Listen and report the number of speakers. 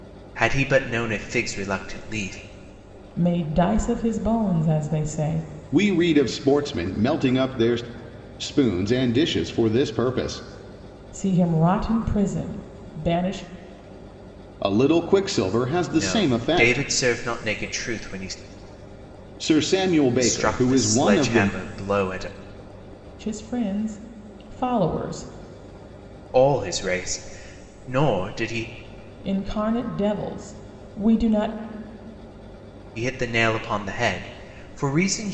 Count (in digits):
3